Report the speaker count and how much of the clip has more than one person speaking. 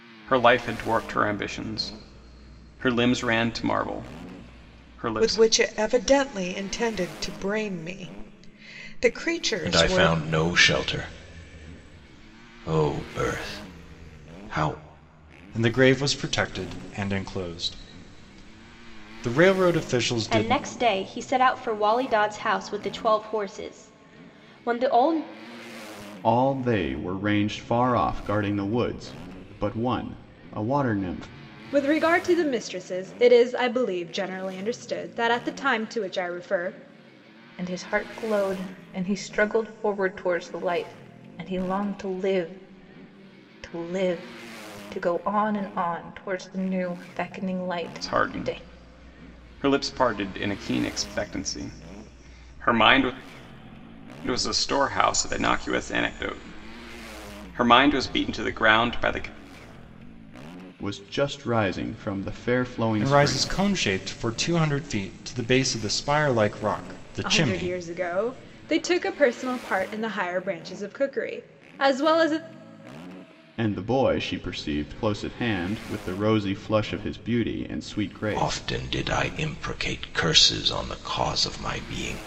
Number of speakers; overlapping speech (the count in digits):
8, about 4%